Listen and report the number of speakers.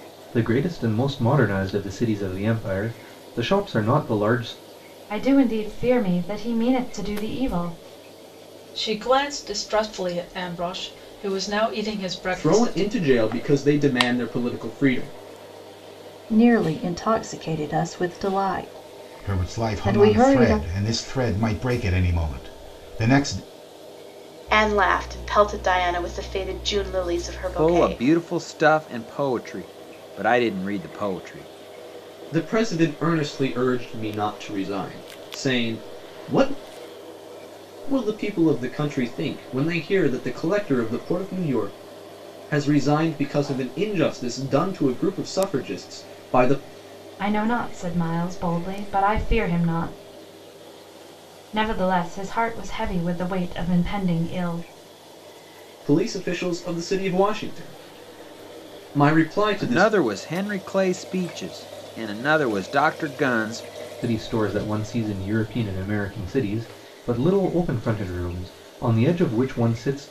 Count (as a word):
eight